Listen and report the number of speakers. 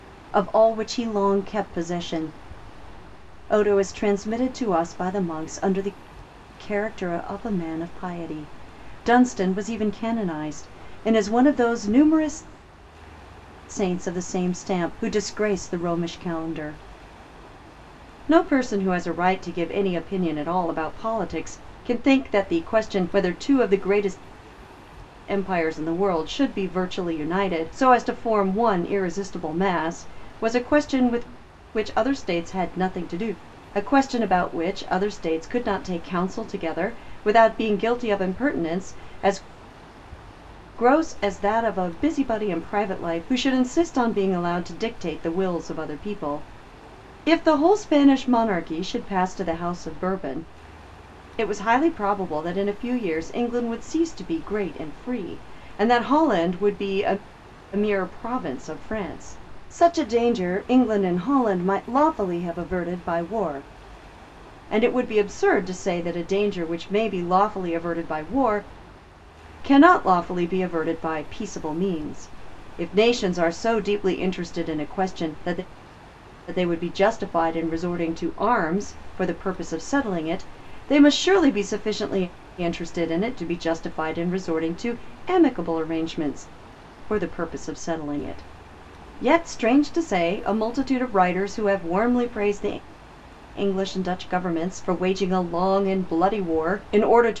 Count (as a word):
one